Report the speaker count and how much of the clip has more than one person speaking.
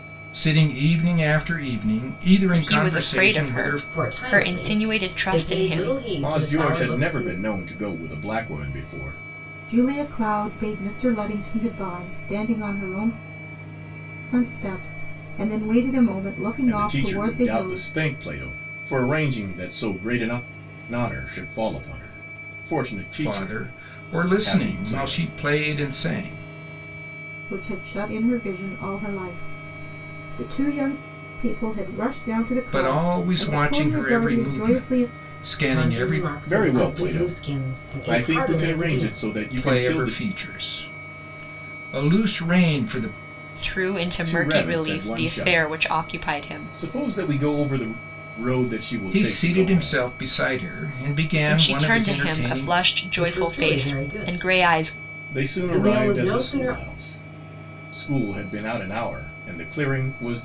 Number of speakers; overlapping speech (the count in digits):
5, about 38%